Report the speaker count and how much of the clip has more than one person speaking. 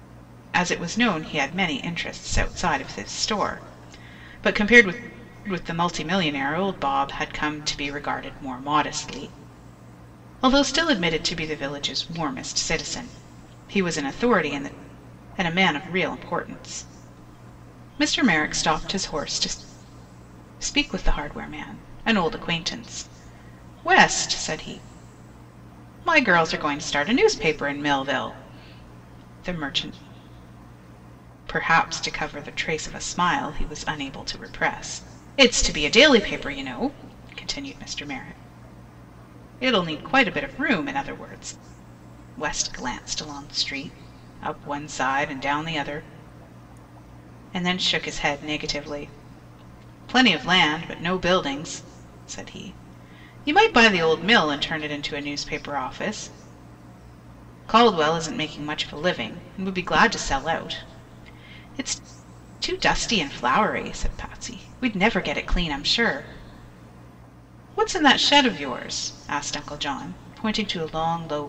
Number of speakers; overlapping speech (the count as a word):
one, no overlap